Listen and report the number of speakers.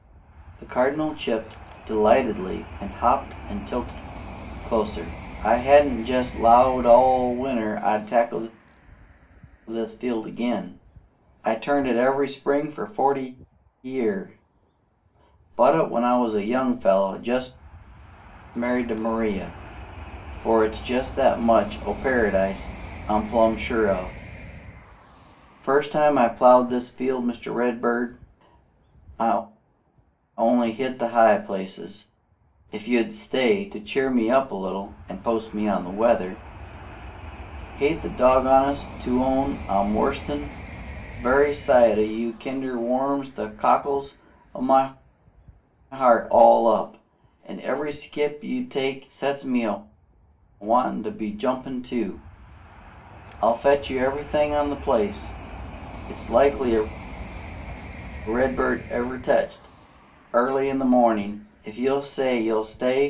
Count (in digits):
1